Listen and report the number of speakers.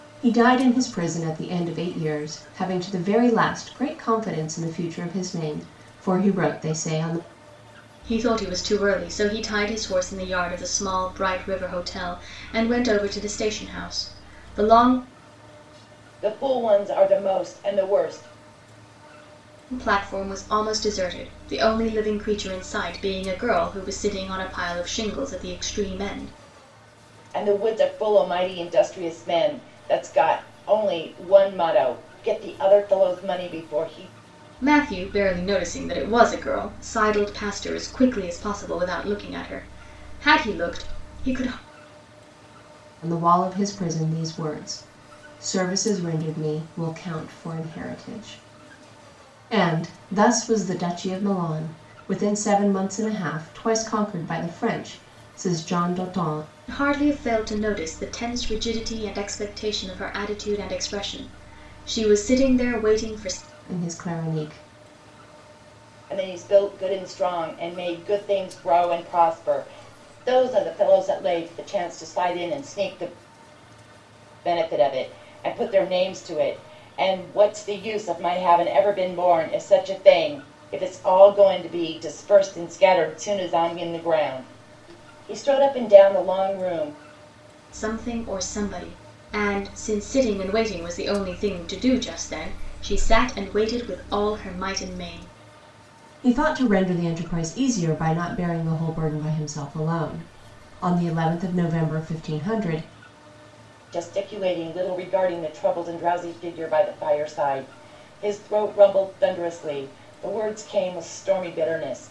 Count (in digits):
3